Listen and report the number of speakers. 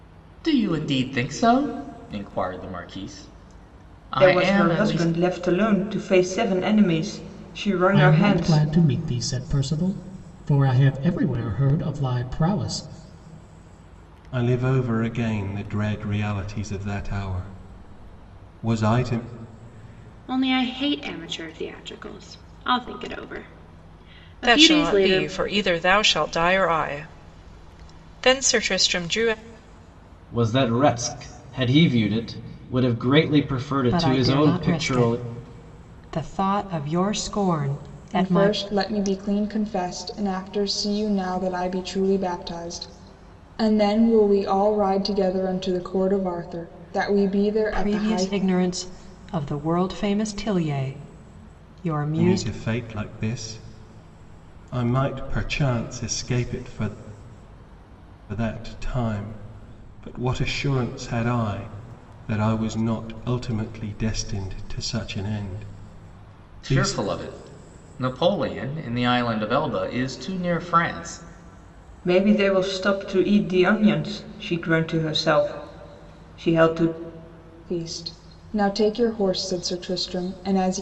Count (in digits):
9